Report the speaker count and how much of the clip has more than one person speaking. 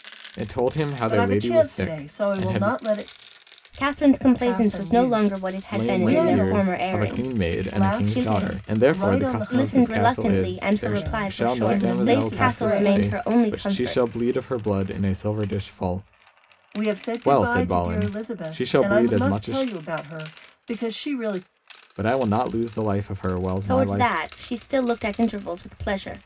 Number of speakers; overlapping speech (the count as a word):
three, about 55%